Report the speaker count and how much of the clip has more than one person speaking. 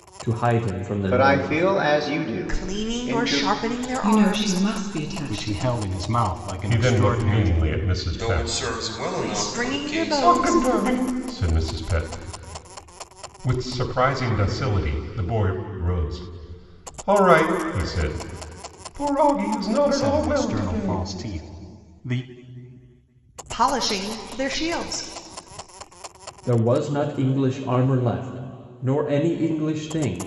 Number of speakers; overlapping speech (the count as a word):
seven, about 24%